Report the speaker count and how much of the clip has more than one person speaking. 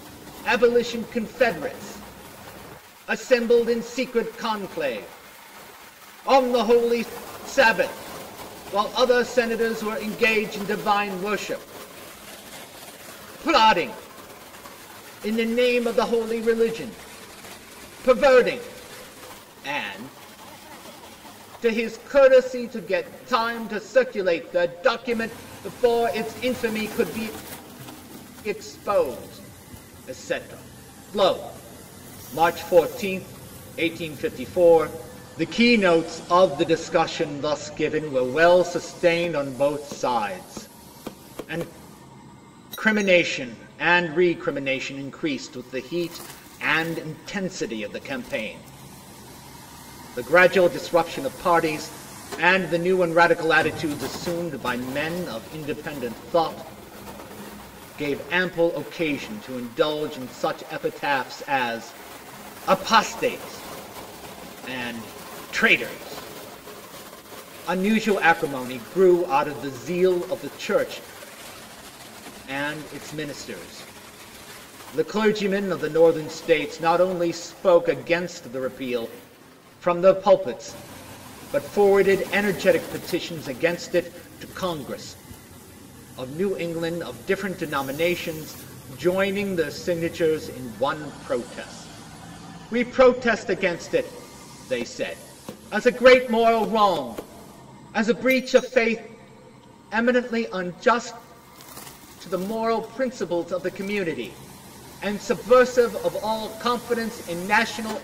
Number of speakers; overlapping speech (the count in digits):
1, no overlap